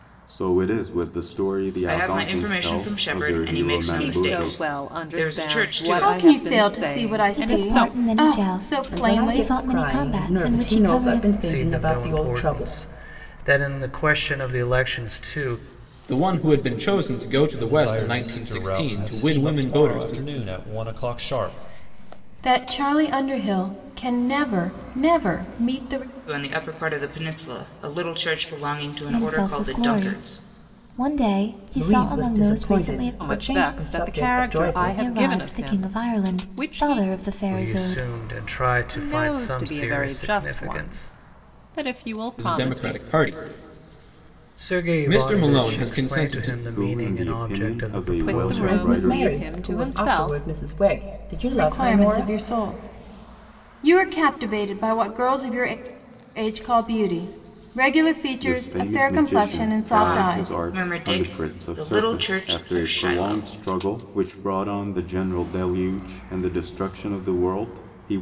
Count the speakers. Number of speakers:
9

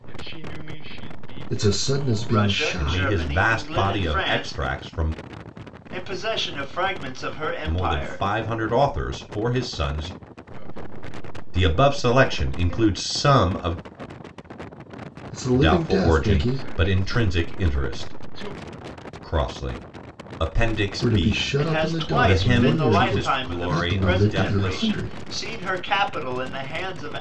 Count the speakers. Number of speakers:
4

